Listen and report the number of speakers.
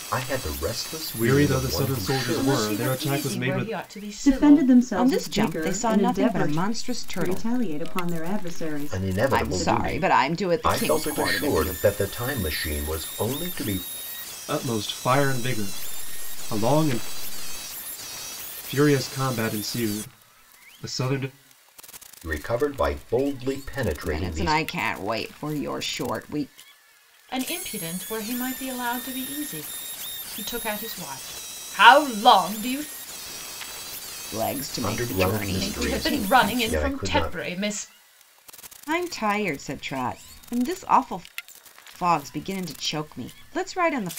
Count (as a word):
six